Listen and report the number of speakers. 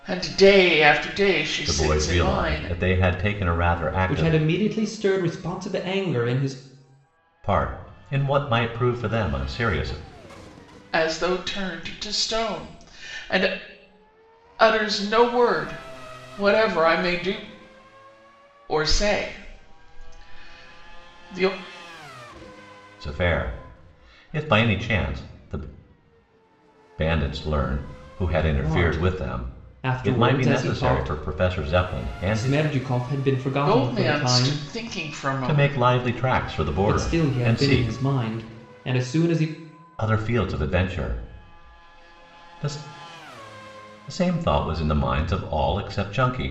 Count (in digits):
3